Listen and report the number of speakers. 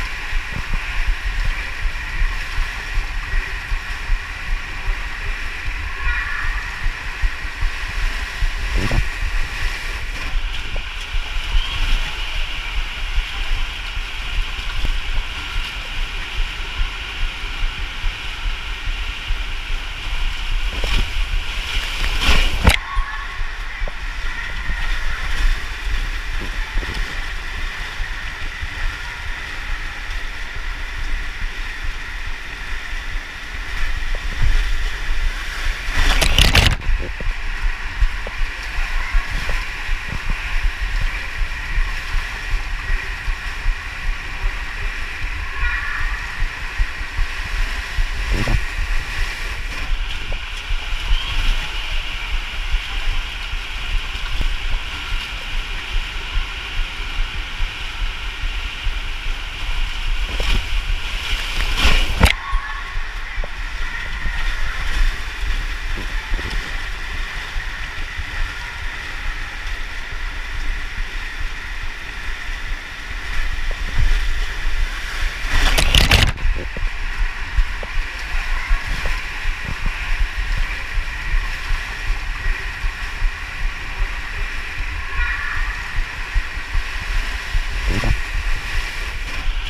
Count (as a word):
zero